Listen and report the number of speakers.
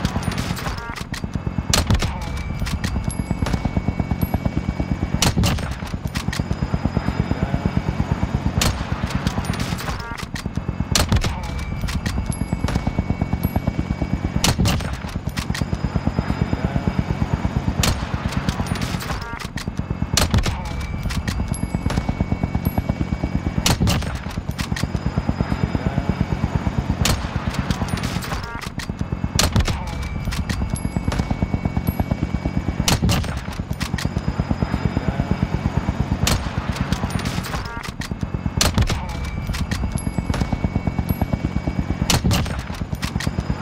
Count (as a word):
zero